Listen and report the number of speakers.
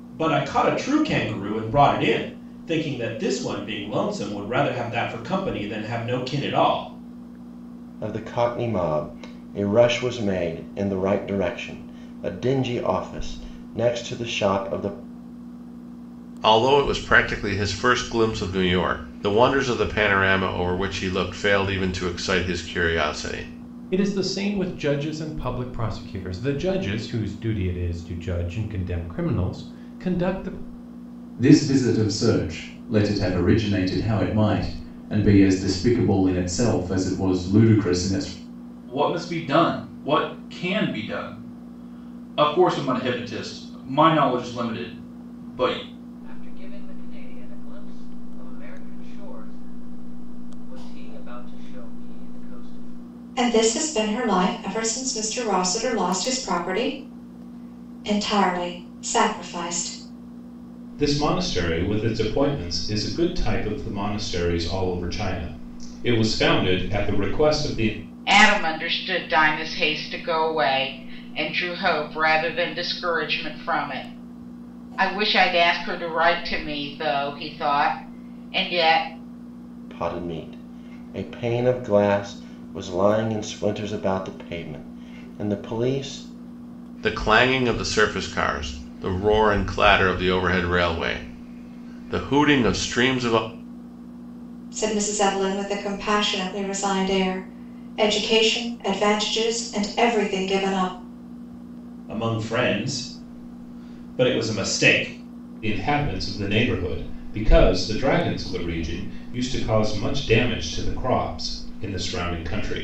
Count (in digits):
10